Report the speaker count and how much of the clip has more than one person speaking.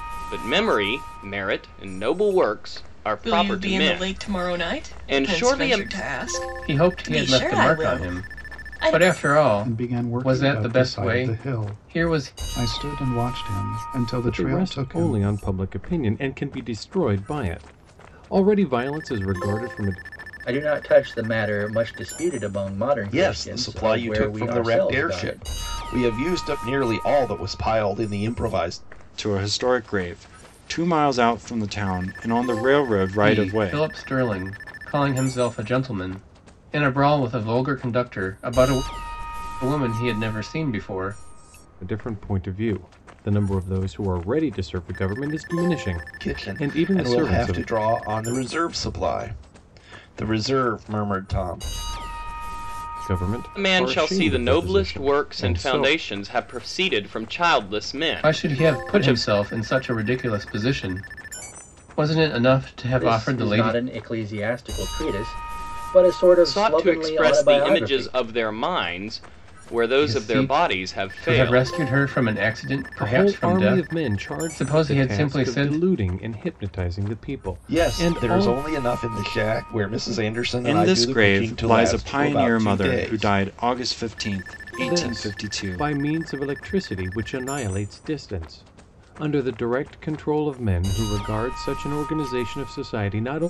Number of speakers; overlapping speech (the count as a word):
eight, about 31%